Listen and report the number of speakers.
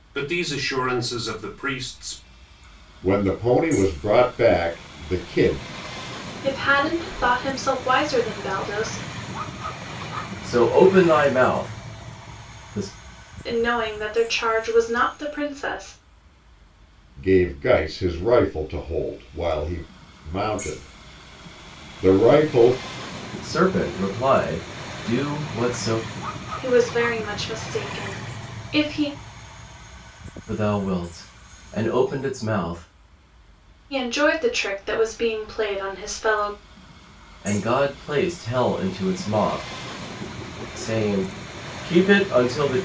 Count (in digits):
4